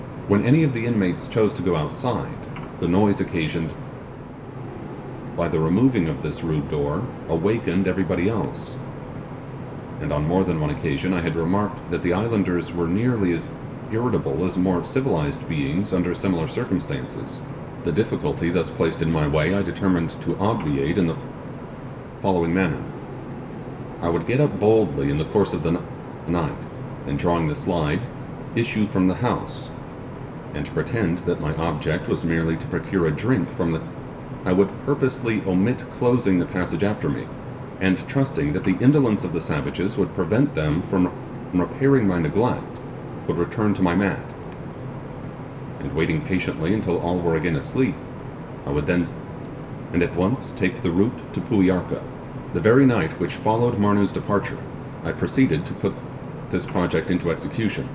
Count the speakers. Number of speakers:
1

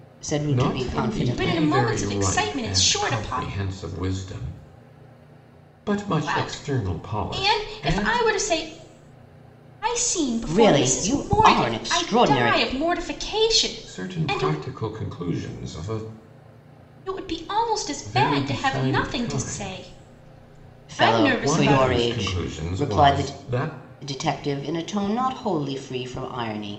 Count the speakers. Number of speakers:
3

